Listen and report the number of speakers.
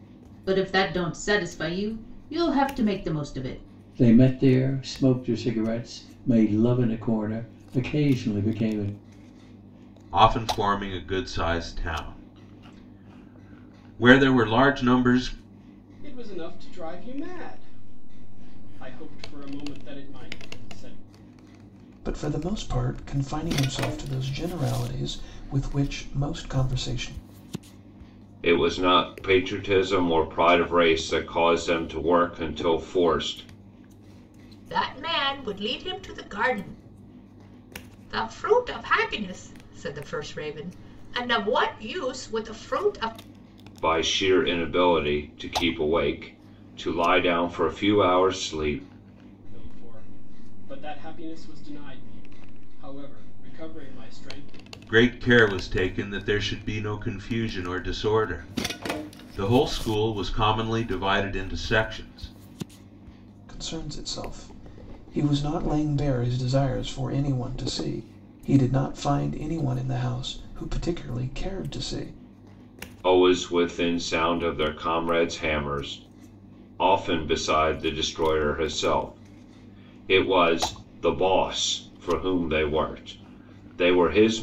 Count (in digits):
7